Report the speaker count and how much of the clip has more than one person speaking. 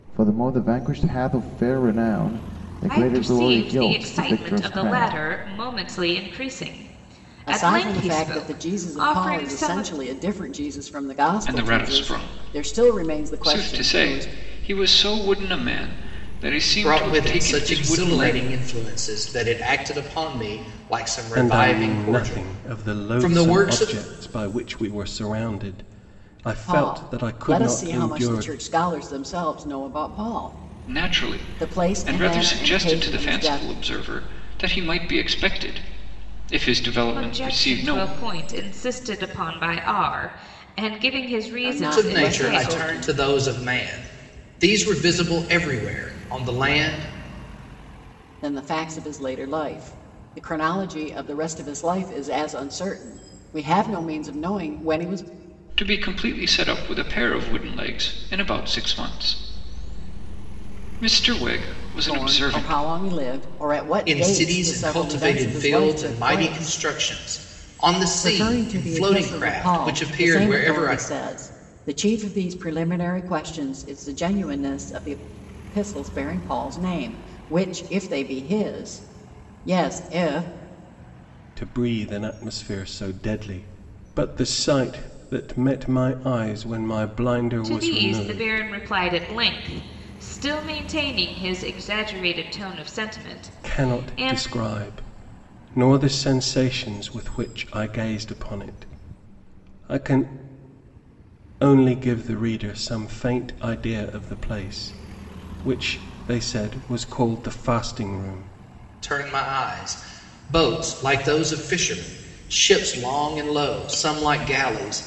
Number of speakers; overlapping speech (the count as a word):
six, about 24%